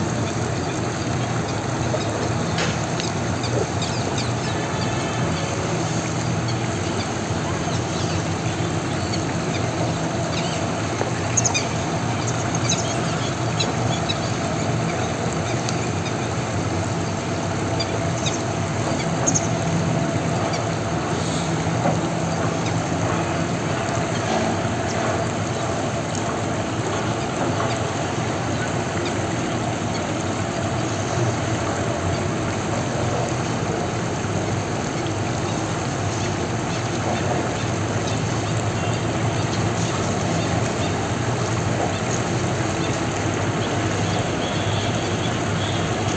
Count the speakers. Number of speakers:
zero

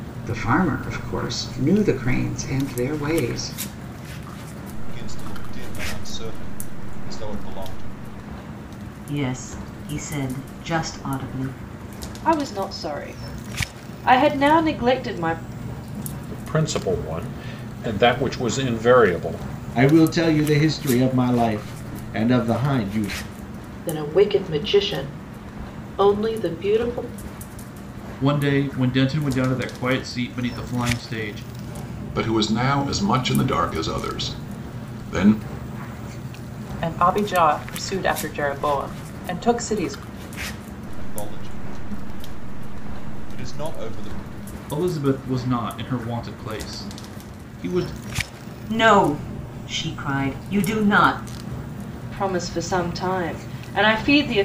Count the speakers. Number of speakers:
ten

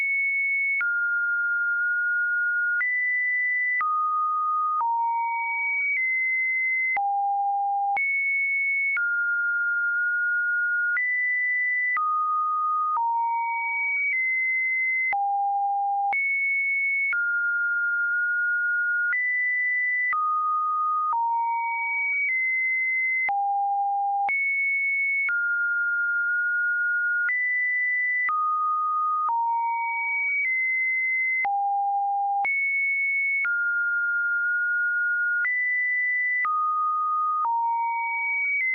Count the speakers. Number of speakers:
zero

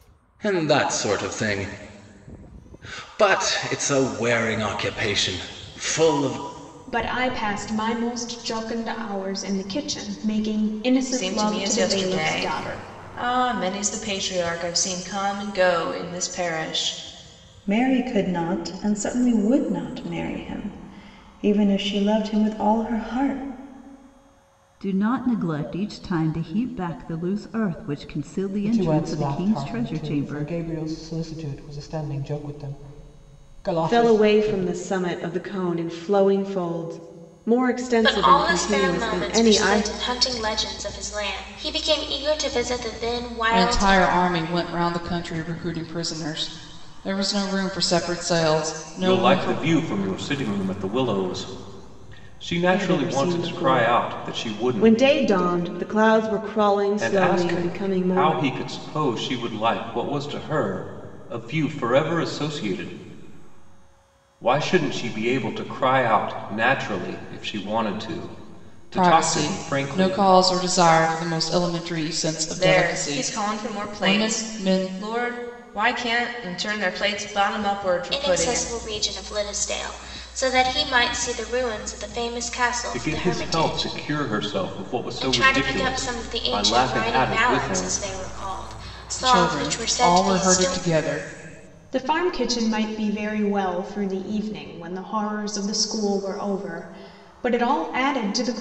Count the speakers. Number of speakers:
ten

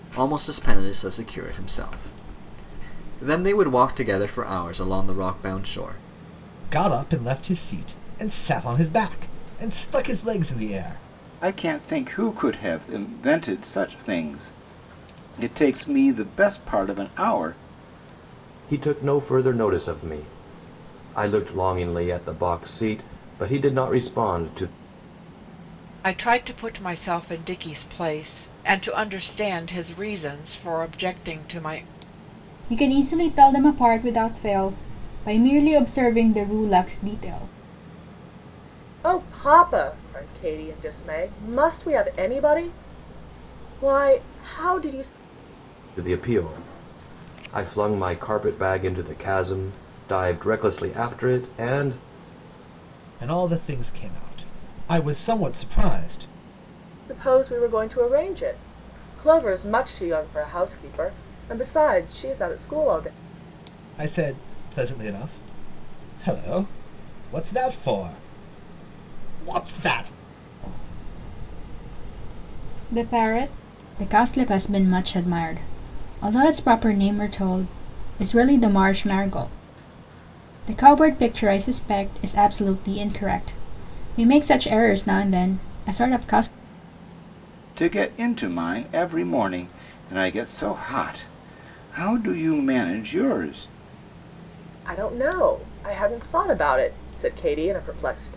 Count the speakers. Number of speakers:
seven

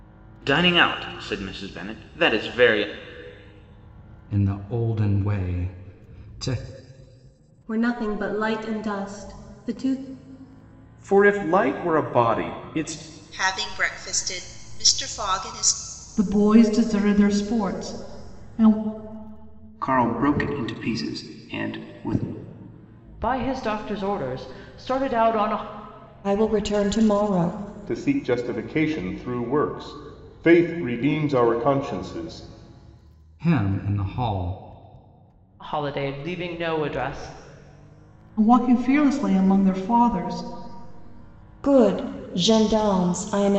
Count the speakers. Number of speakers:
ten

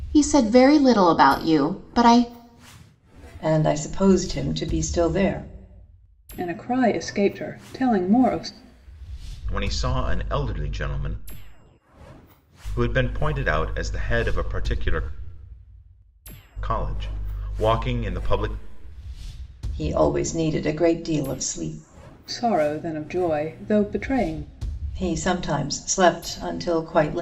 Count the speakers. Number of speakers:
four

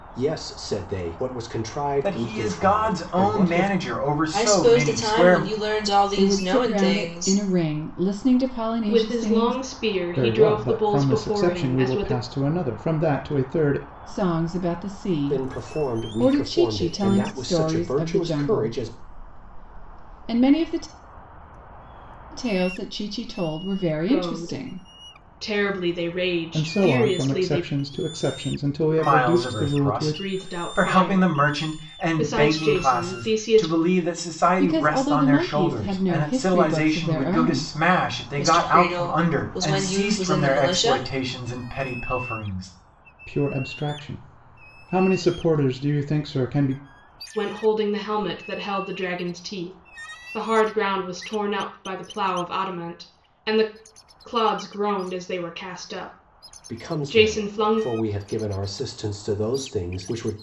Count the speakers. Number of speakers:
six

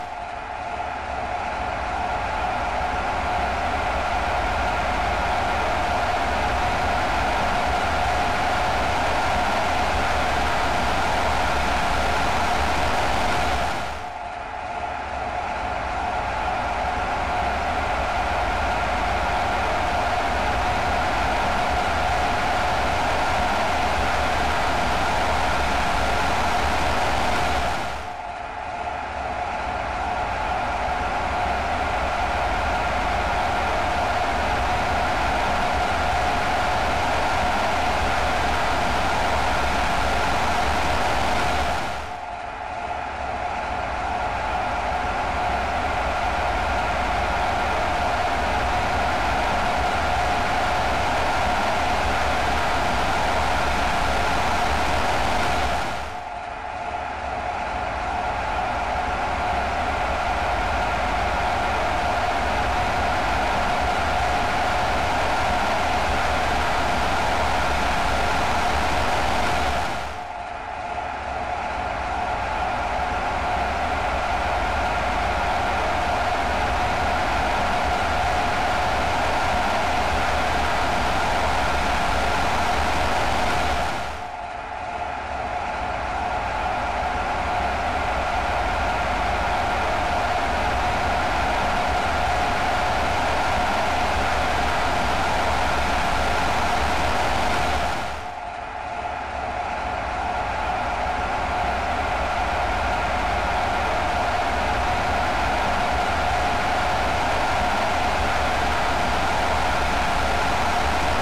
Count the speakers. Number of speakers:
zero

